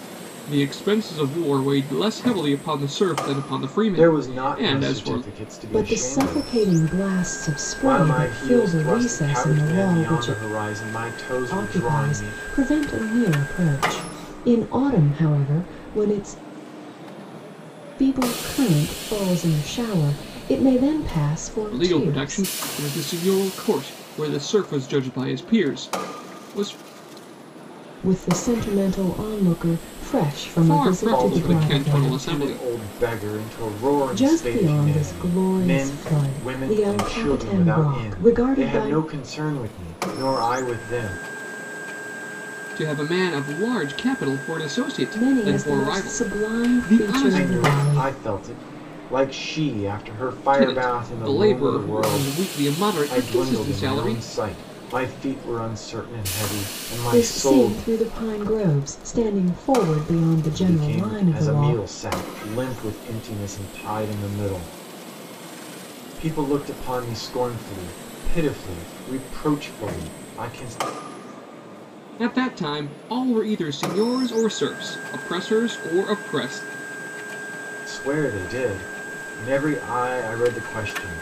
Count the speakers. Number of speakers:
3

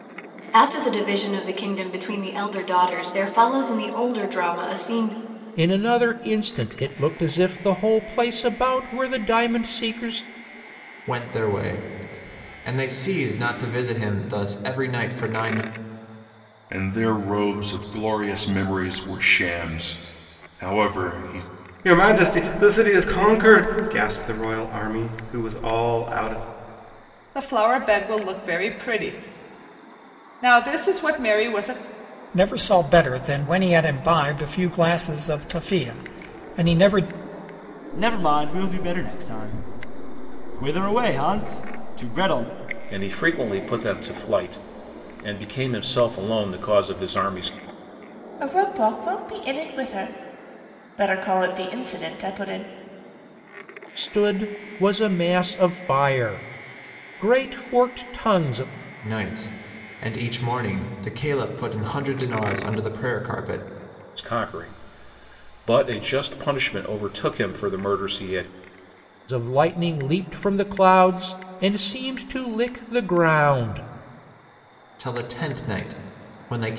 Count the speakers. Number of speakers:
10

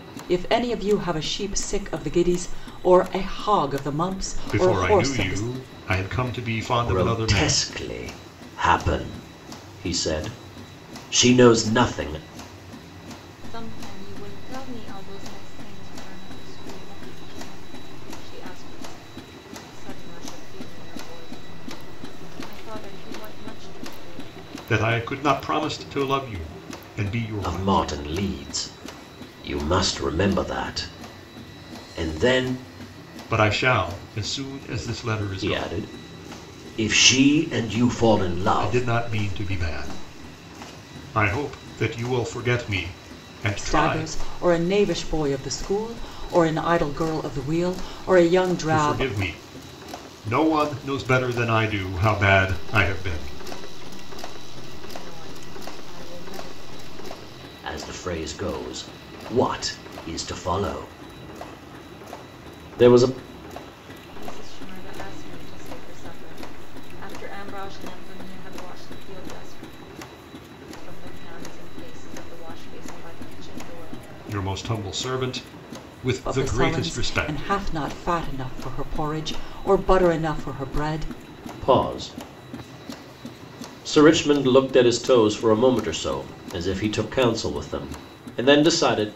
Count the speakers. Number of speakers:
4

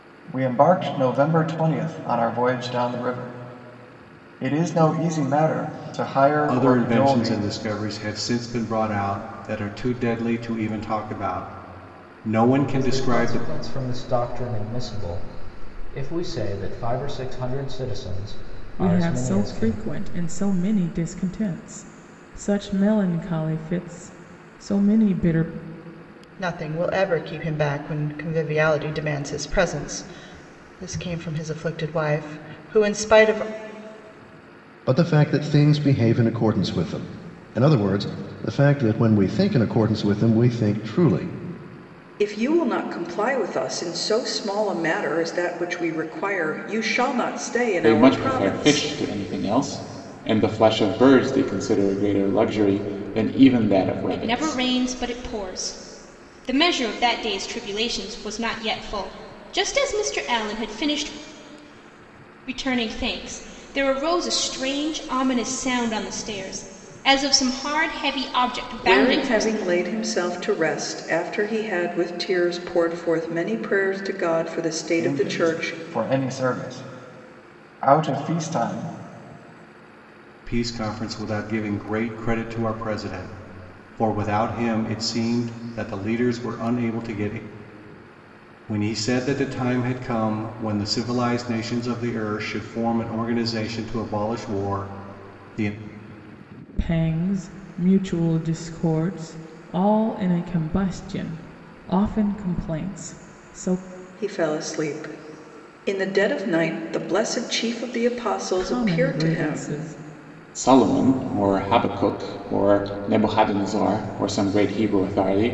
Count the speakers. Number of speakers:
9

